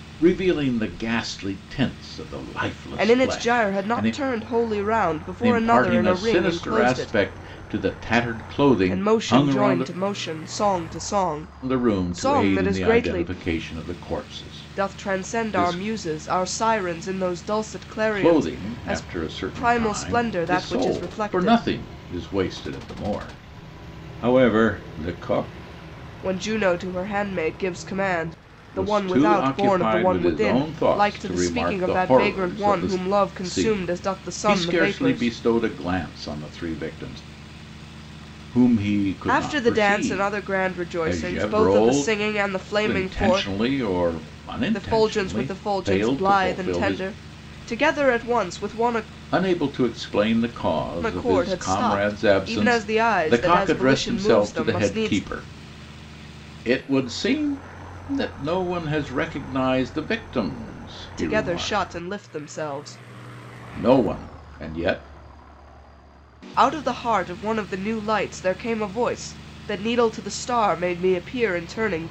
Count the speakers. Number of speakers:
2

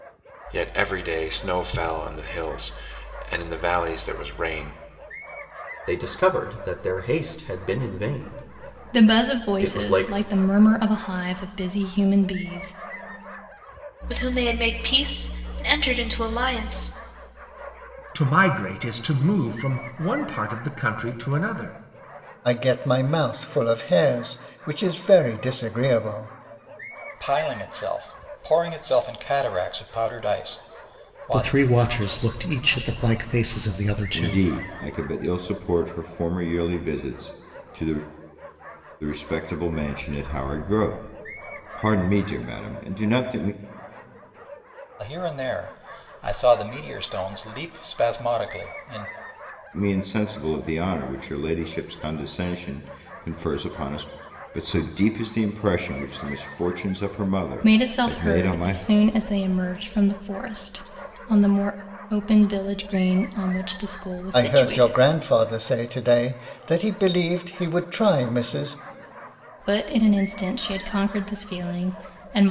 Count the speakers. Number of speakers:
9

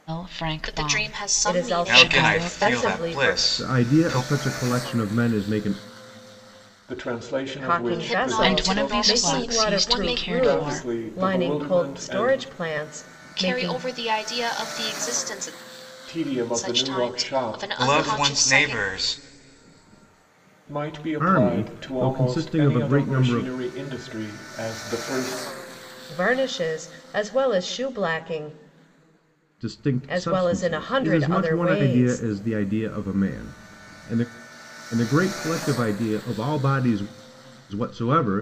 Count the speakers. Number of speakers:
6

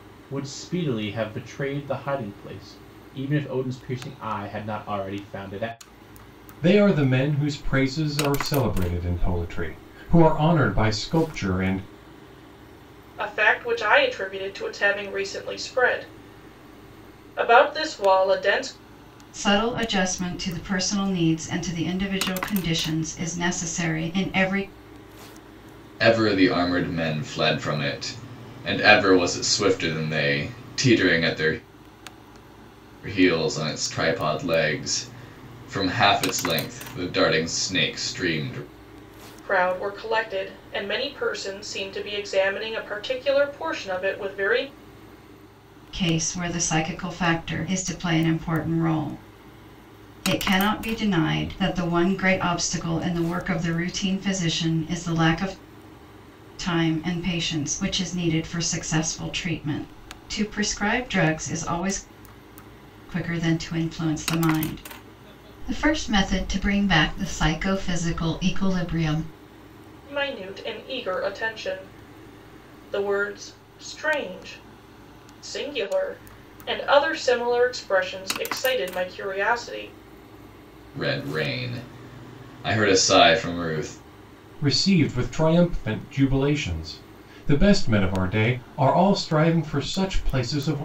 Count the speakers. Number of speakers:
5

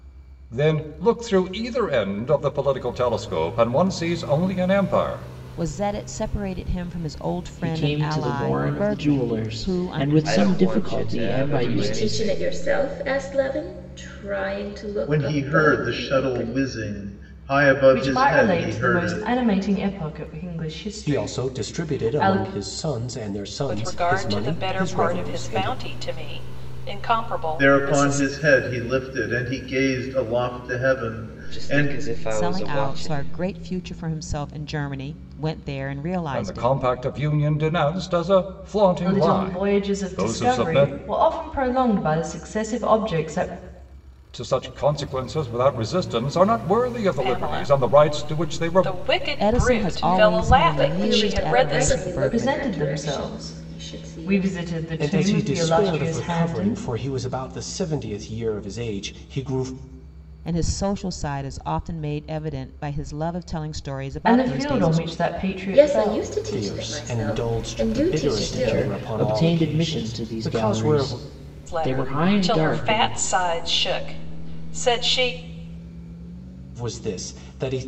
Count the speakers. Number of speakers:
9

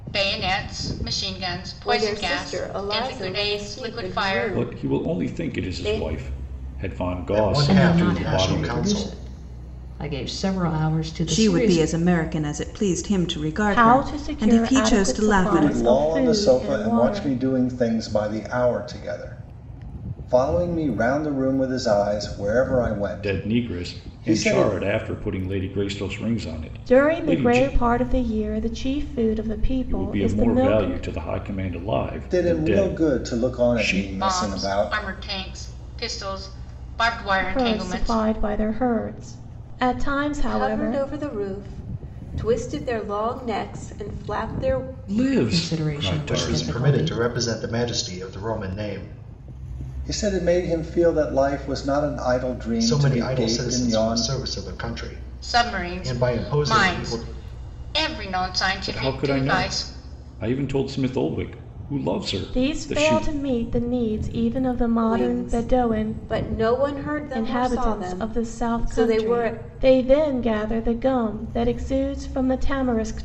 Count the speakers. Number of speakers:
8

